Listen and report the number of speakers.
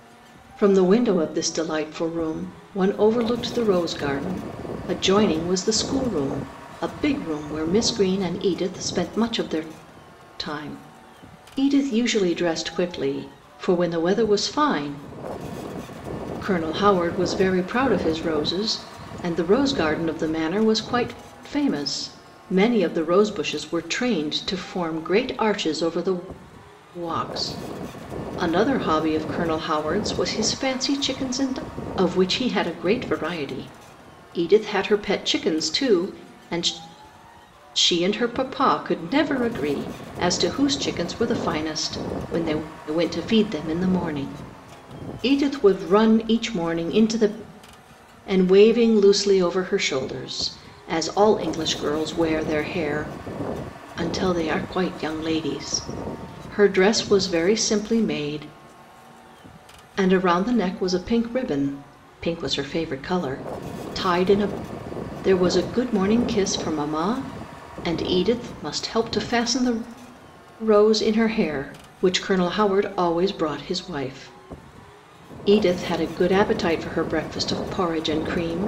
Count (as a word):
one